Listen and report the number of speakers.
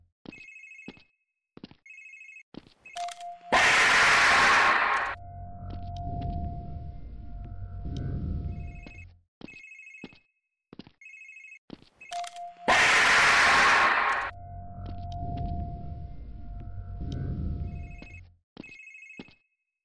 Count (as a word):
zero